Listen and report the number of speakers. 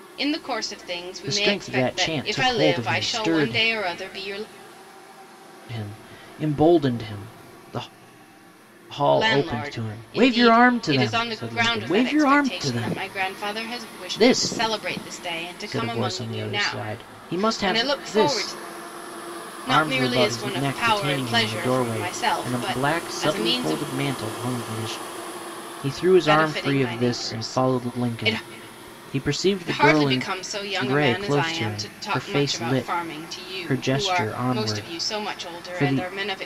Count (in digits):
2